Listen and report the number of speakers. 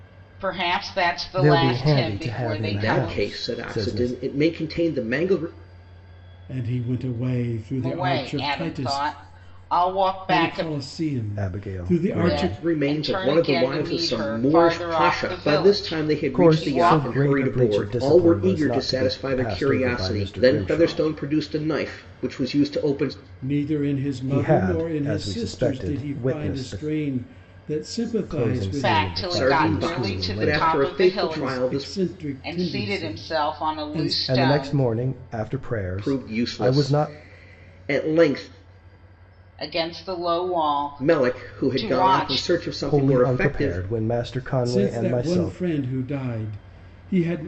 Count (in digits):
4